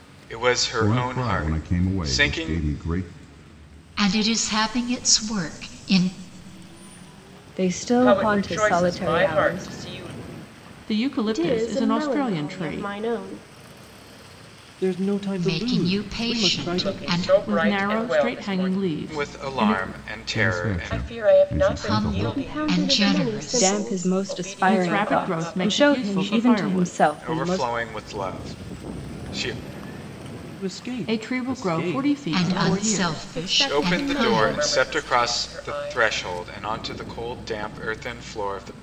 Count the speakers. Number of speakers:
eight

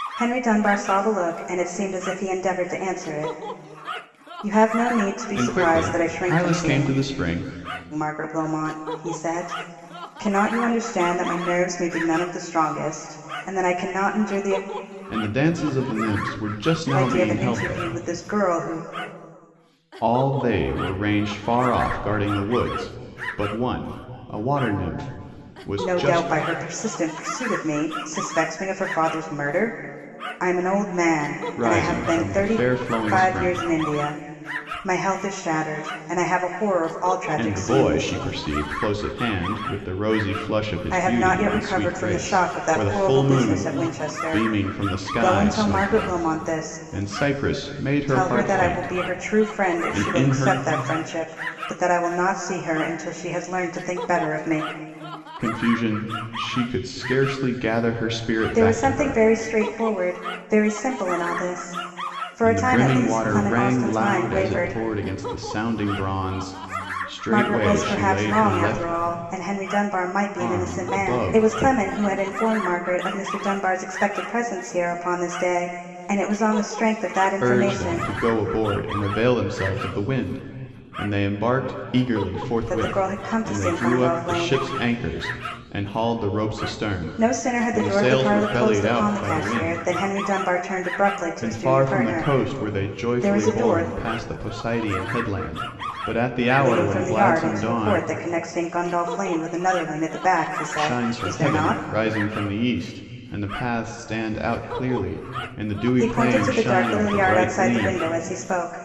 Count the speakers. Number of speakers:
two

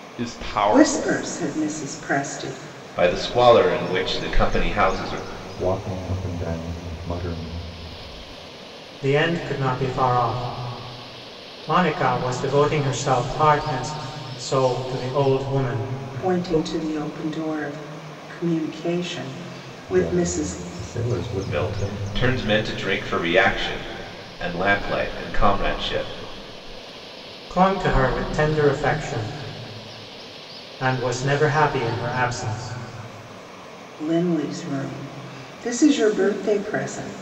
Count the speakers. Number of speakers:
five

